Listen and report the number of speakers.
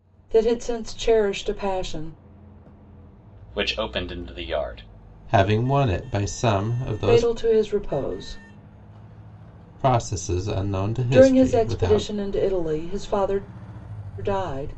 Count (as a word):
three